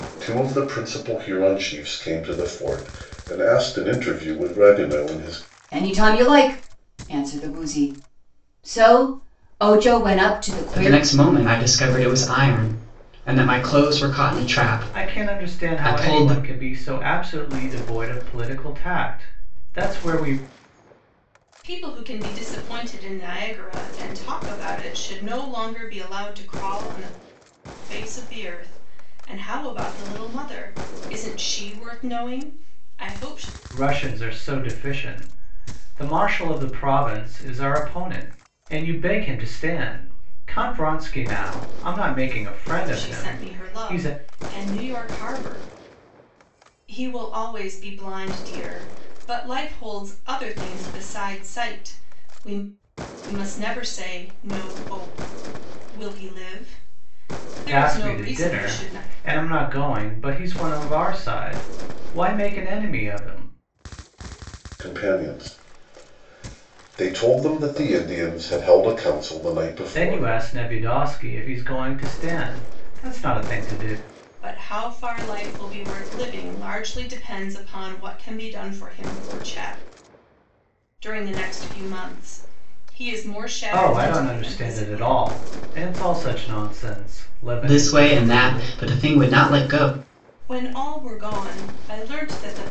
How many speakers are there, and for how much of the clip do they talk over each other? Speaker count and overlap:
5, about 8%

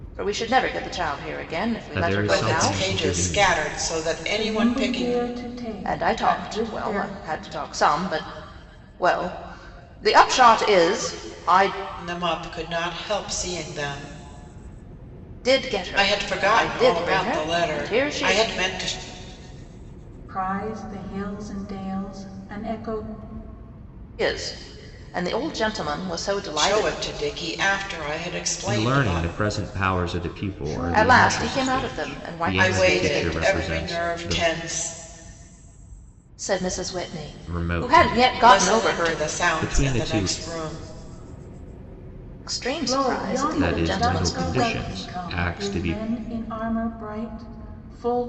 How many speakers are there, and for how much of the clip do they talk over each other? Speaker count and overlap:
4, about 36%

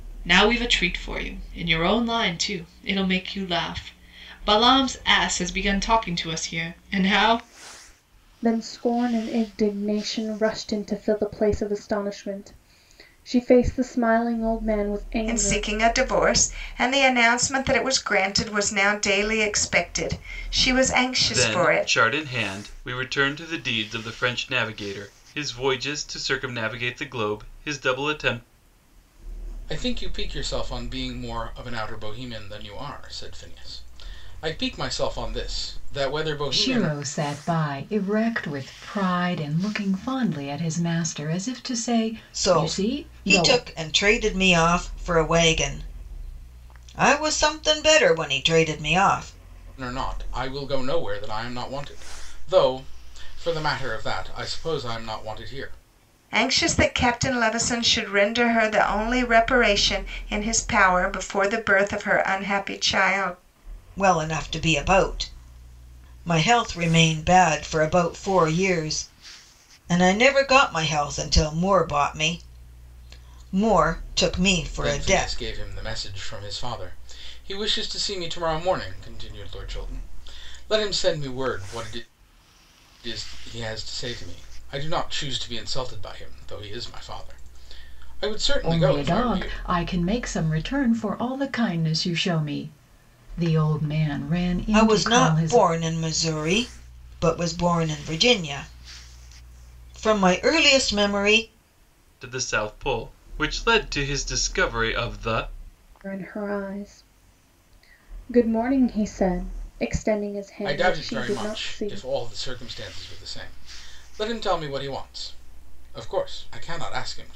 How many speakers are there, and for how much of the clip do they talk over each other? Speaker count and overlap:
7, about 6%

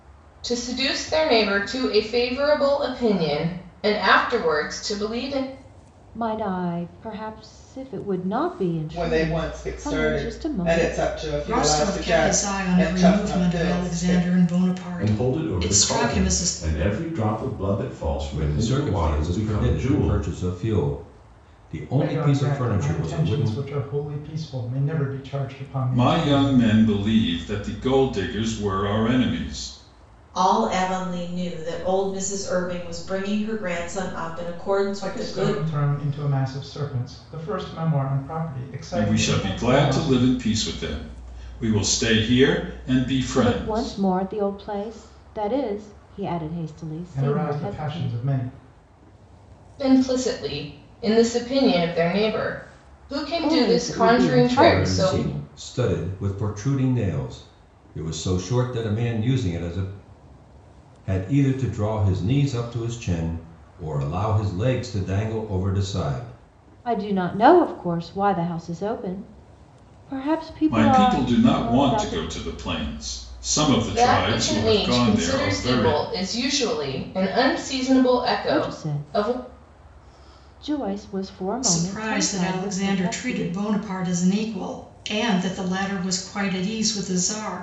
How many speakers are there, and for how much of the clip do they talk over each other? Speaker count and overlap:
9, about 27%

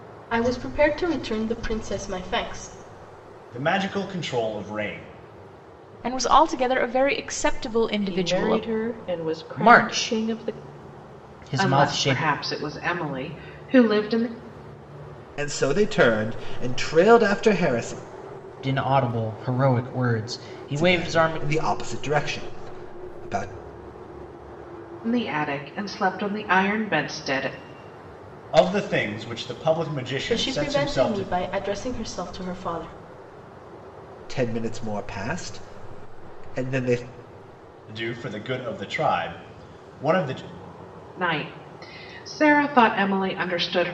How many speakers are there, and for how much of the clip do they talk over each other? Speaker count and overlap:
7, about 10%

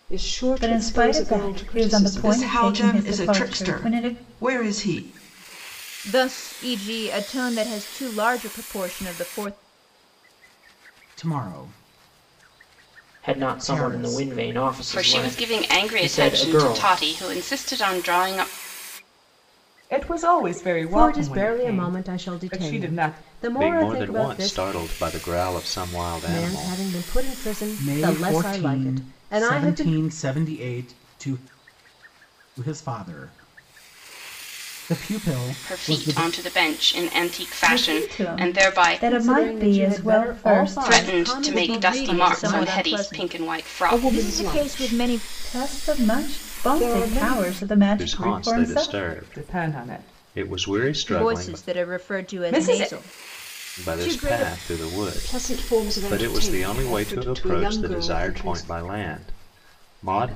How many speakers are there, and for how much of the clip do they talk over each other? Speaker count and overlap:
10, about 53%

